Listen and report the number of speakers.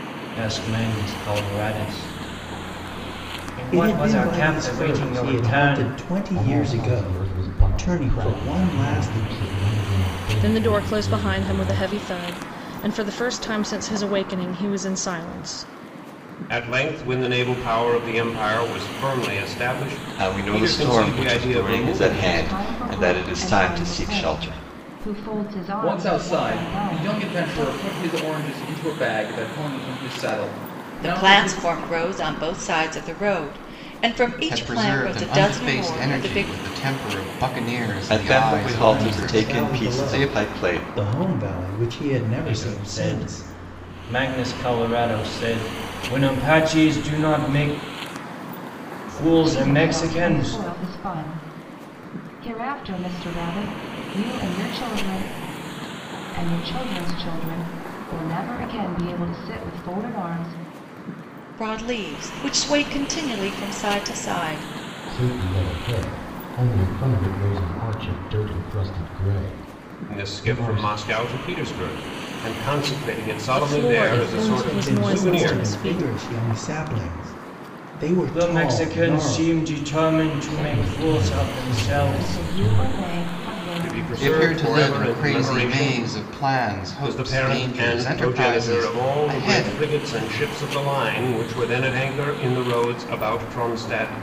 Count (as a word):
ten